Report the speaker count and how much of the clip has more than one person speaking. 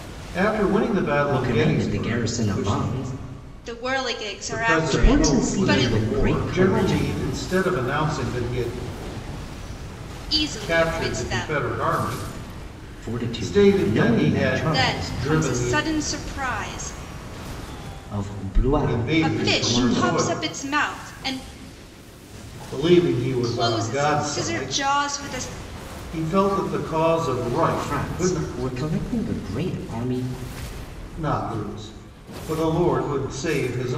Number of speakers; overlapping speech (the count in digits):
3, about 34%